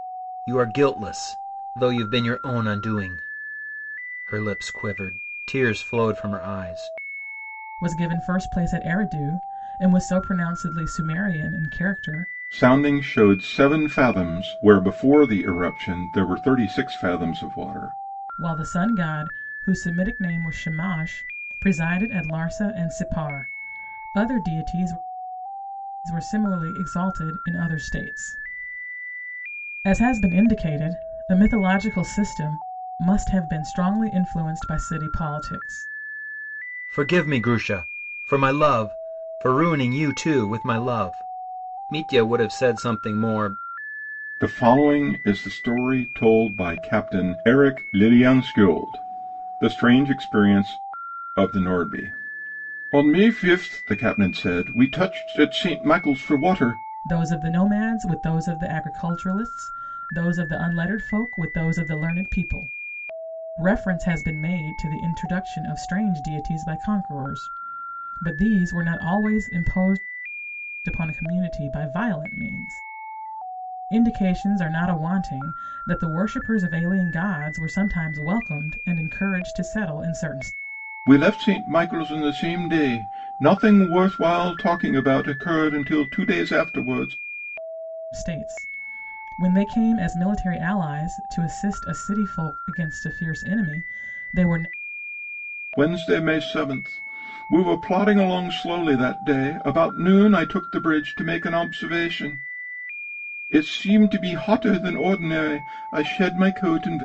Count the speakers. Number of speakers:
three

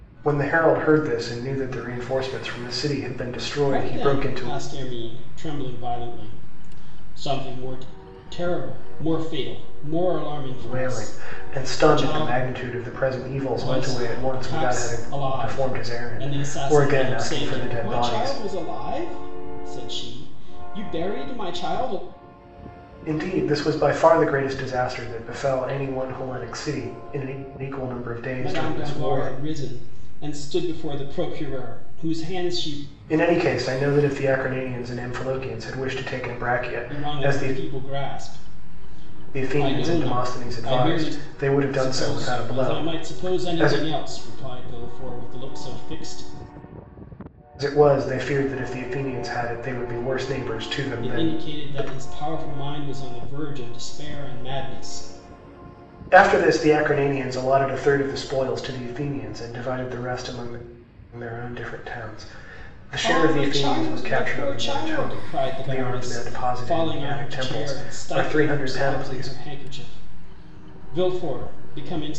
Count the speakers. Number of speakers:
two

